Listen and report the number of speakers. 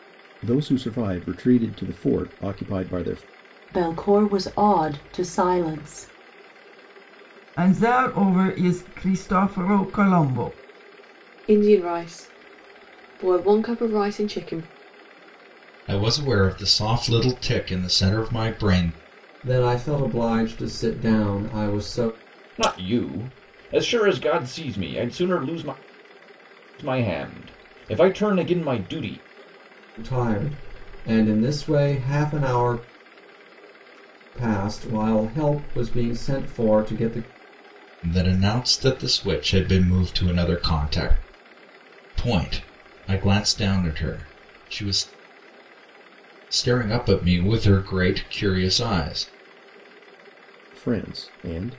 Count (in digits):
7